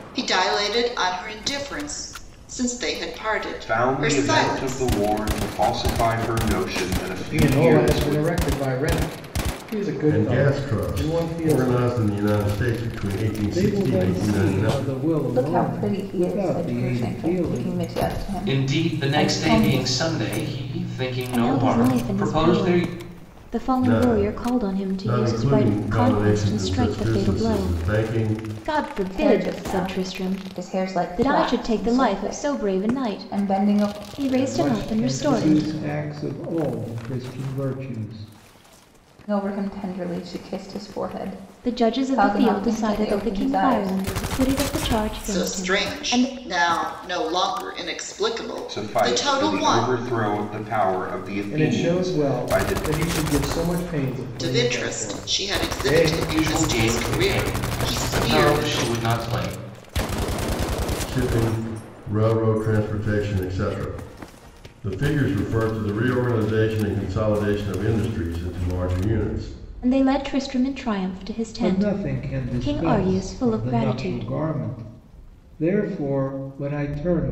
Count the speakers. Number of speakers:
8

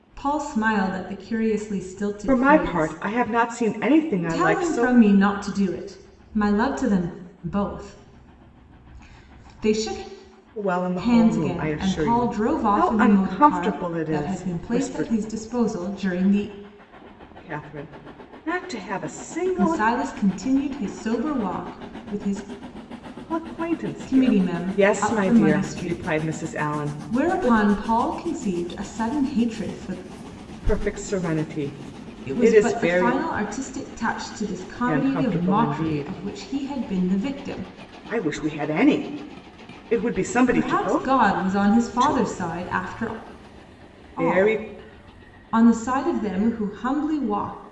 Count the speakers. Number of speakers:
2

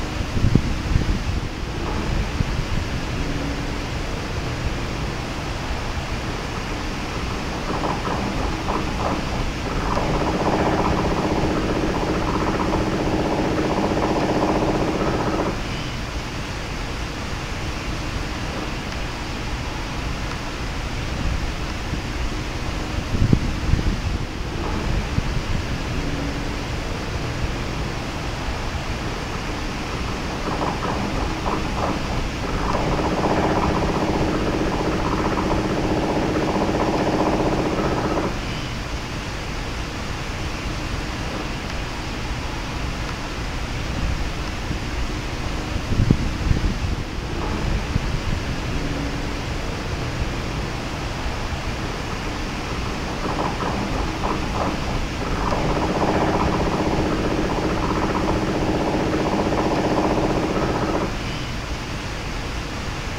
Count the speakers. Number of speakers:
0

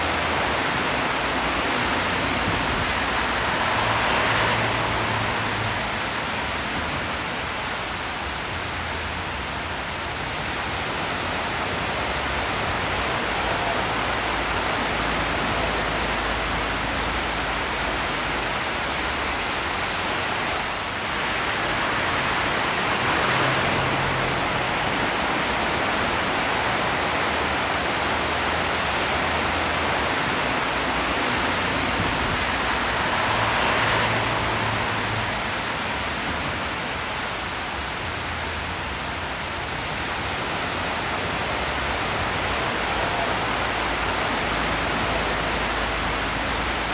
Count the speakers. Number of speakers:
0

